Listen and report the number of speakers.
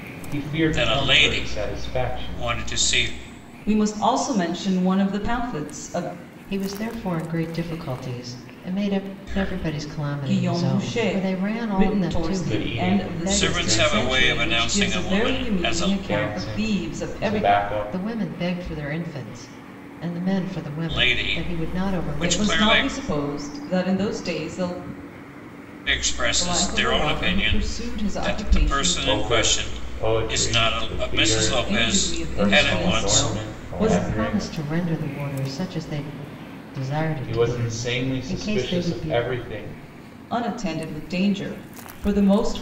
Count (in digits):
4